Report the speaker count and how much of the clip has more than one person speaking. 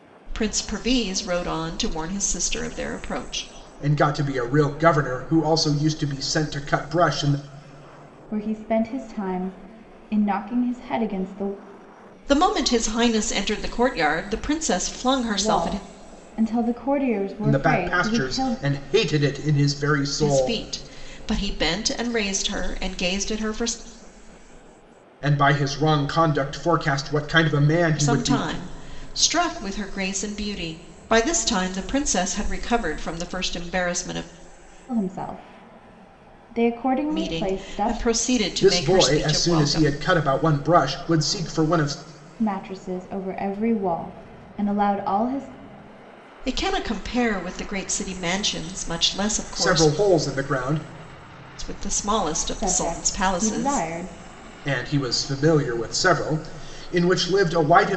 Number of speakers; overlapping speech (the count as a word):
three, about 12%